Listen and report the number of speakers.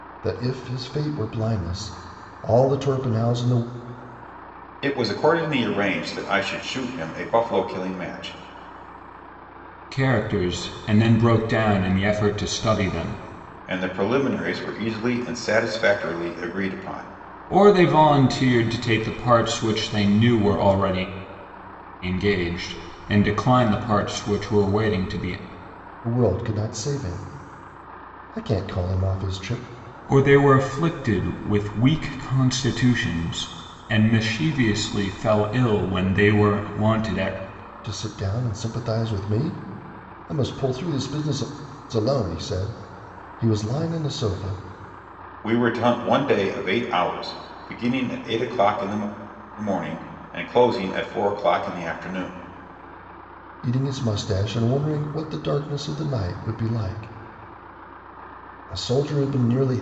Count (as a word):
three